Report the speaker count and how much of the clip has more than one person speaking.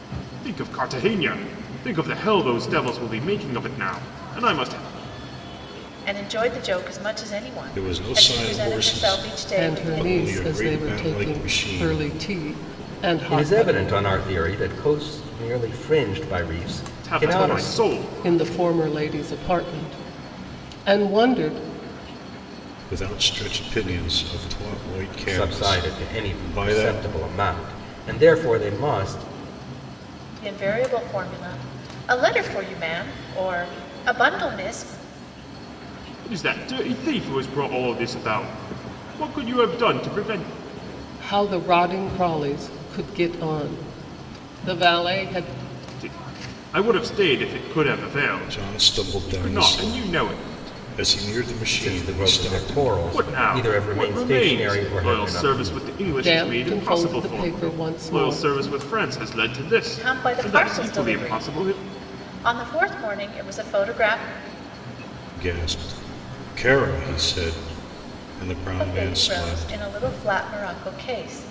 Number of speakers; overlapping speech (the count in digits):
5, about 27%